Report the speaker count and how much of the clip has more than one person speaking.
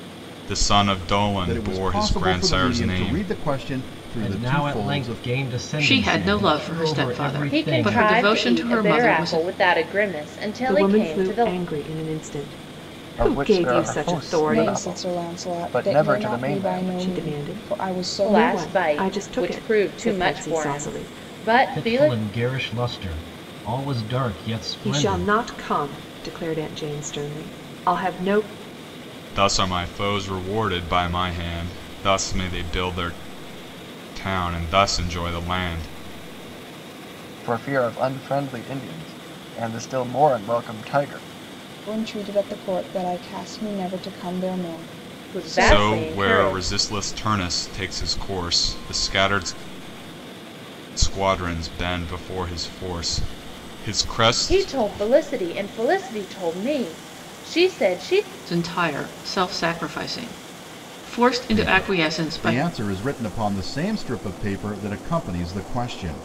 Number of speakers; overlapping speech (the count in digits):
8, about 30%